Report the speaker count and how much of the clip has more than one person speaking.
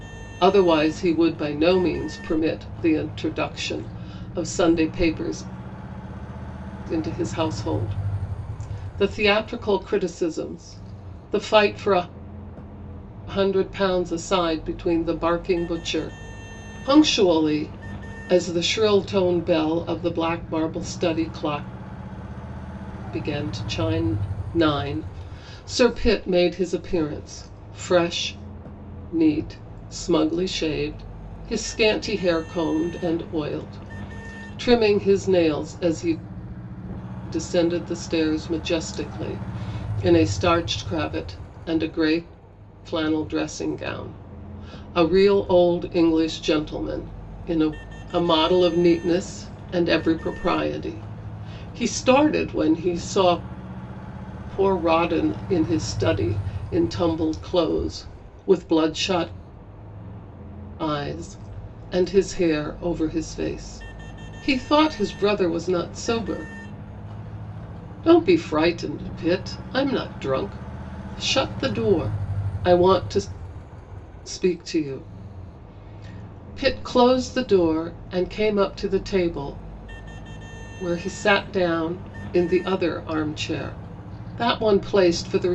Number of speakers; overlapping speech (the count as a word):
one, no overlap